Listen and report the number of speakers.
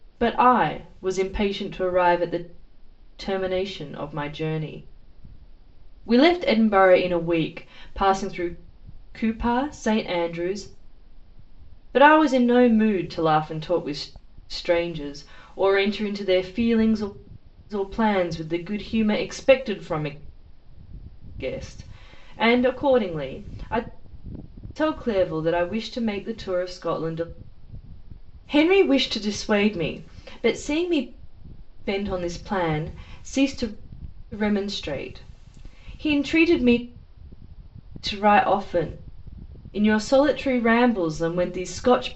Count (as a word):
one